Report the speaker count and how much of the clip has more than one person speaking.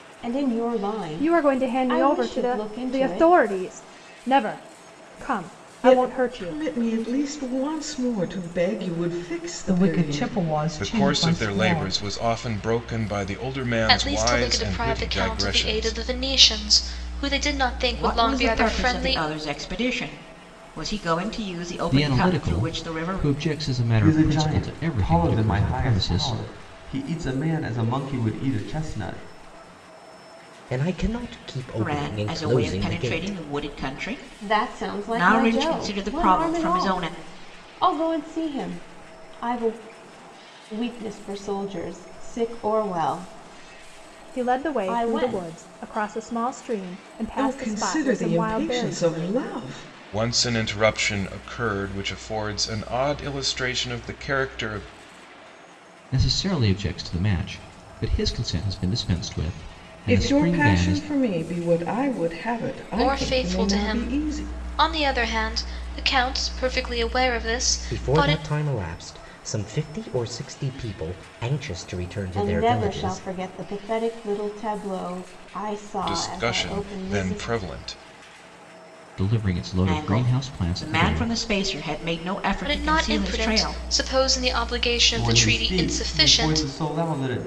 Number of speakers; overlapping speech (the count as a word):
ten, about 34%